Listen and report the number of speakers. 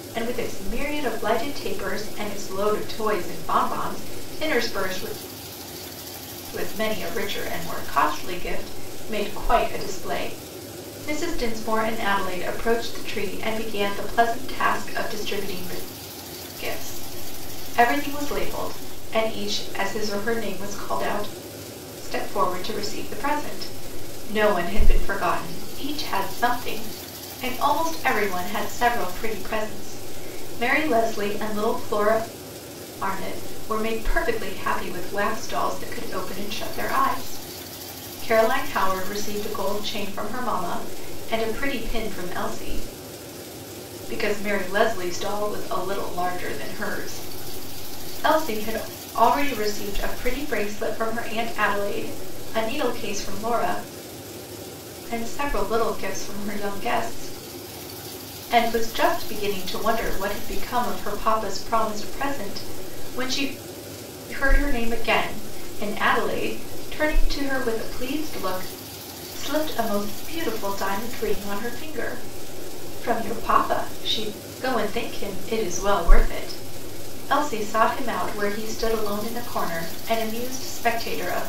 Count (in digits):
1